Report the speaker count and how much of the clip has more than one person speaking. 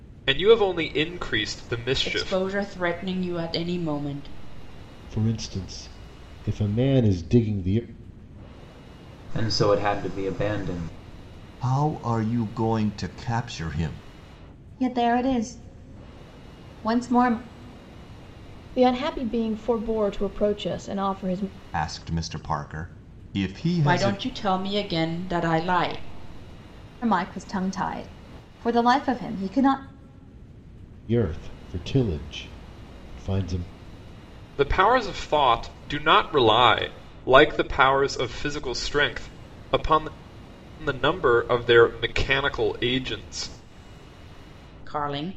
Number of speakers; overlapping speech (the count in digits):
7, about 2%